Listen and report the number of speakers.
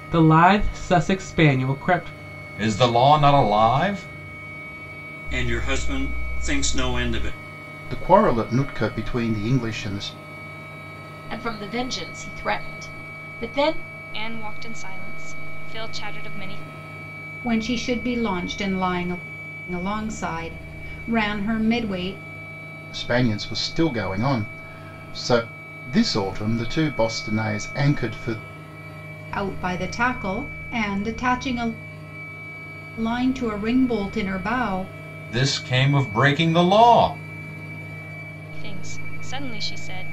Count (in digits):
7